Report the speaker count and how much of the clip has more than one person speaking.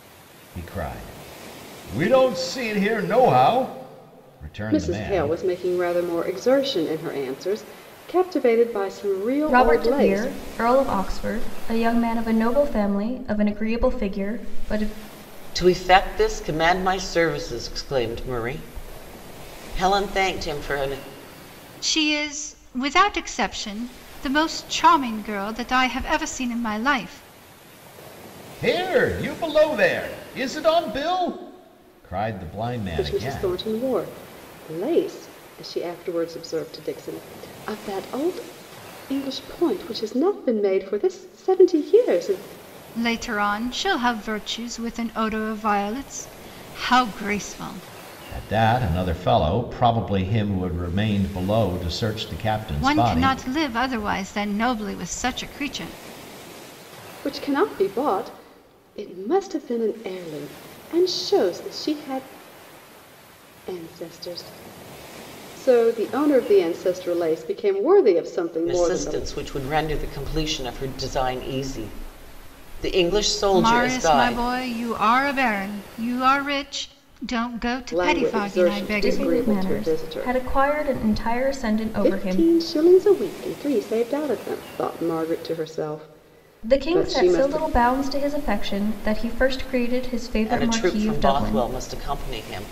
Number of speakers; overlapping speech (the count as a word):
five, about 10%